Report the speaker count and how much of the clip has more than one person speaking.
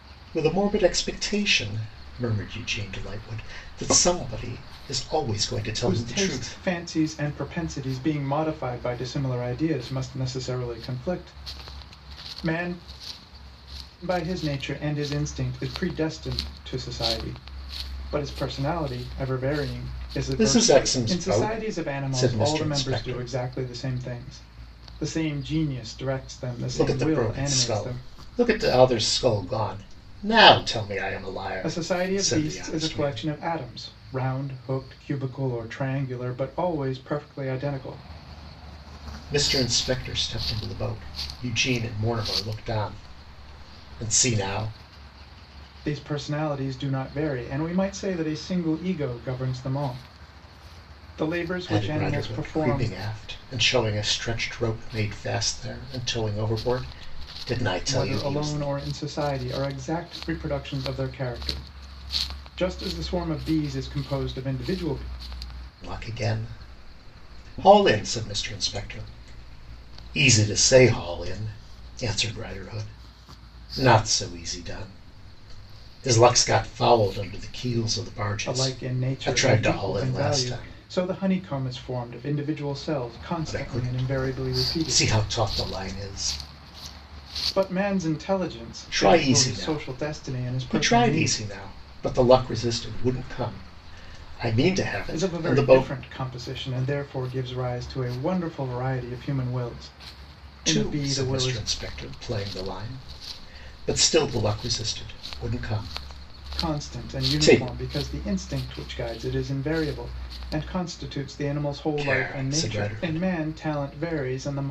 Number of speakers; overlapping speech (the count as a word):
two, about 18%